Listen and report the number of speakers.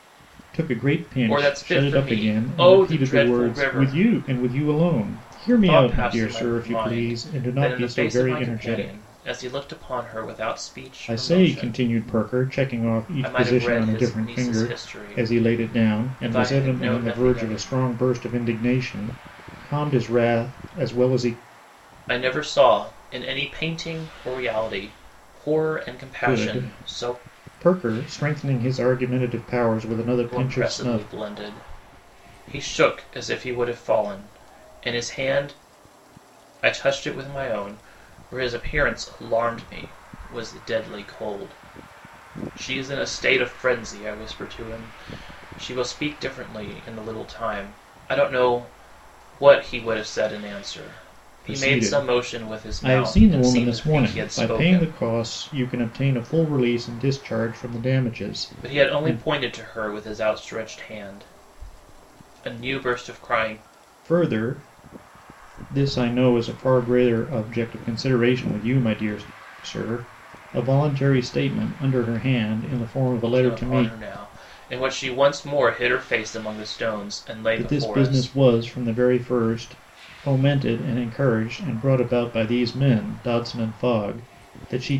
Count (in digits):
2